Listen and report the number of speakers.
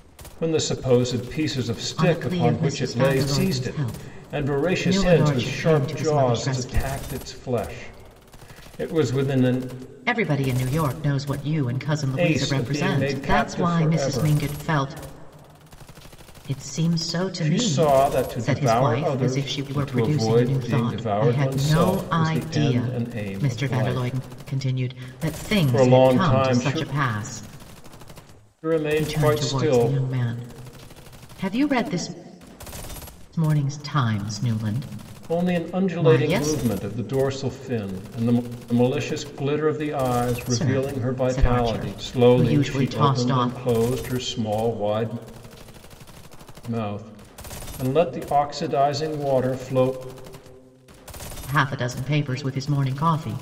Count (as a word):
two